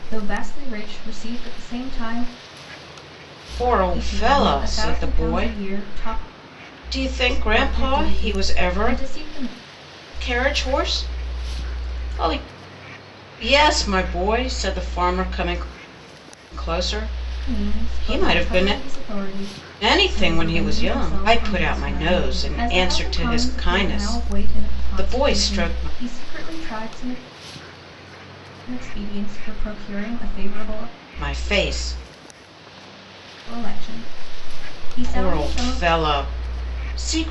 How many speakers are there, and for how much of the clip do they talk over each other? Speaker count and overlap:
two, about 30%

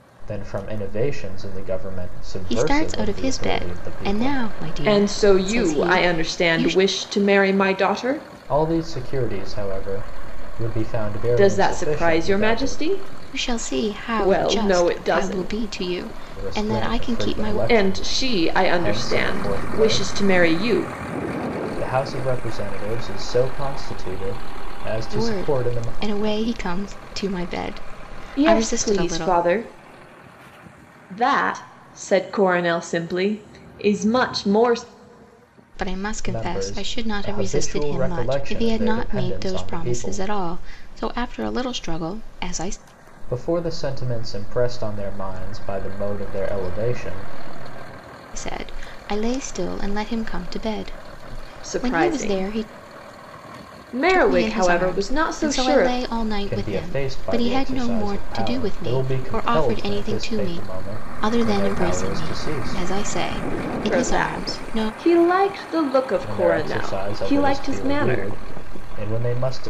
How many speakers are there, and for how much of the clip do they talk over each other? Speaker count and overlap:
three, about 42%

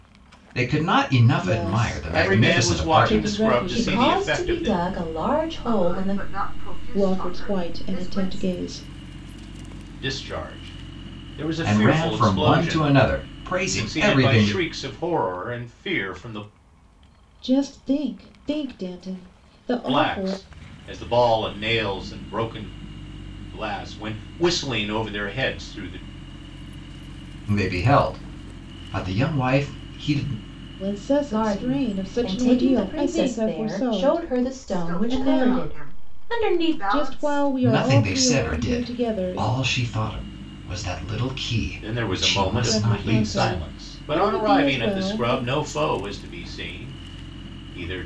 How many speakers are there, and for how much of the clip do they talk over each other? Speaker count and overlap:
five, about 42%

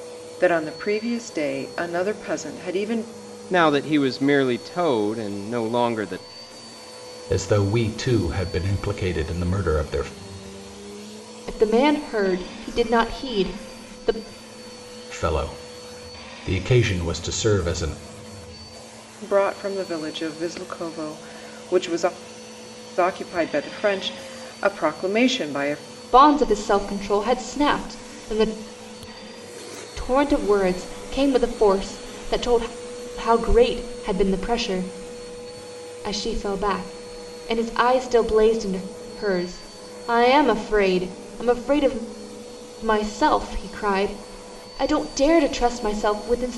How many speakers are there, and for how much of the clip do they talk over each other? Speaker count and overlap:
four, no overlap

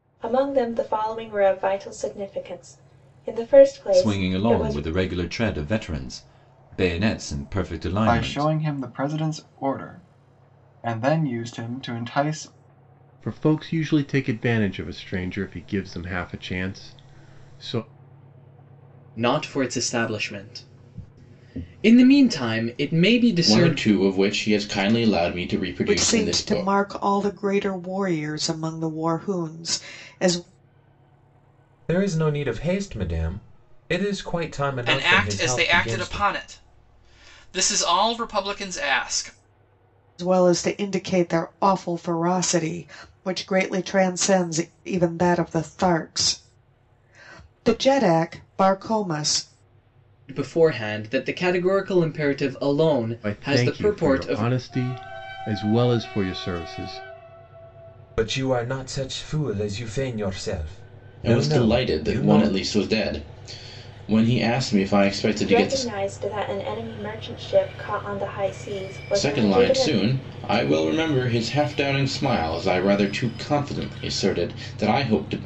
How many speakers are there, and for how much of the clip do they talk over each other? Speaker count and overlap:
nine, about 11%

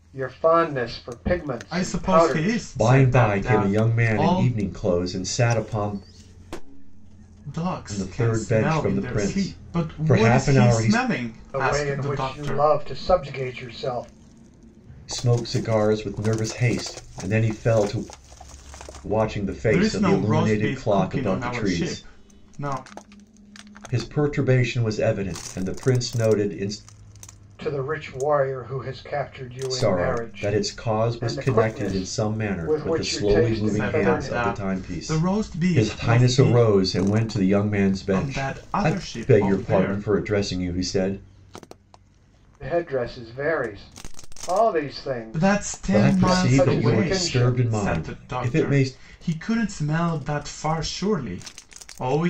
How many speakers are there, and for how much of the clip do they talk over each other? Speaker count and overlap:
three, about 40%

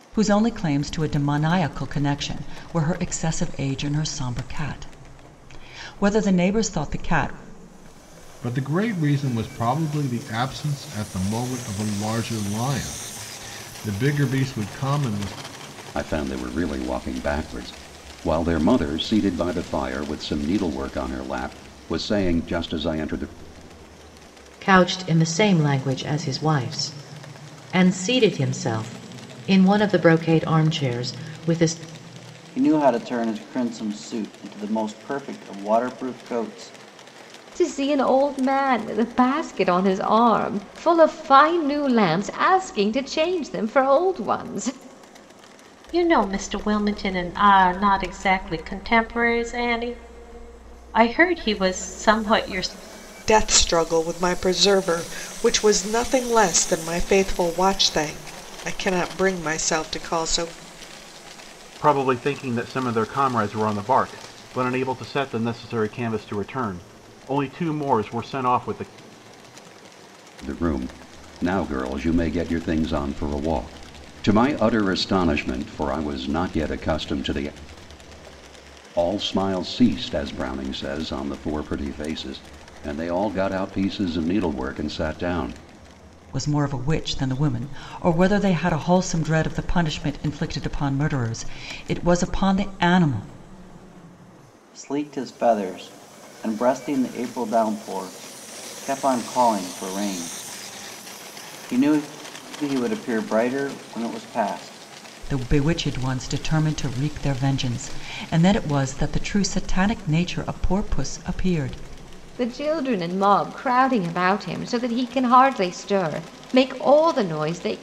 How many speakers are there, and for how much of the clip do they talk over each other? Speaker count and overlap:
nine, no overlap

